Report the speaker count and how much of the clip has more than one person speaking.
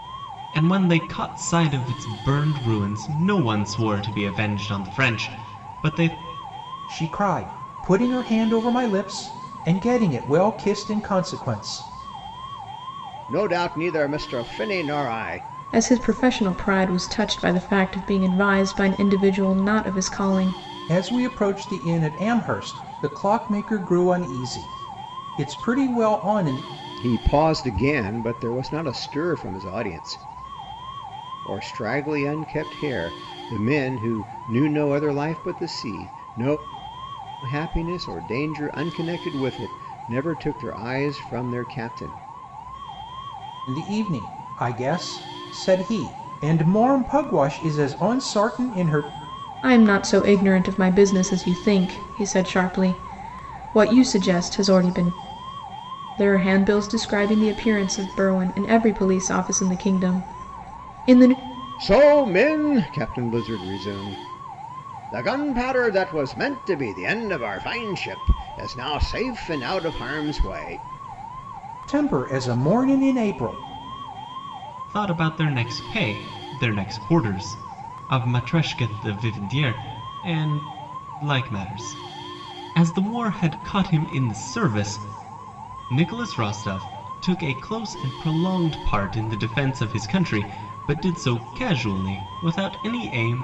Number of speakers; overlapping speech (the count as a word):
four, no overlap